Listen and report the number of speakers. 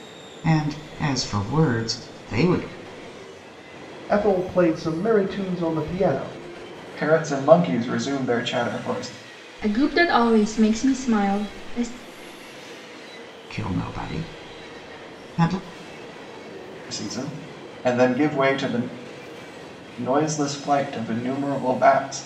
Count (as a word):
four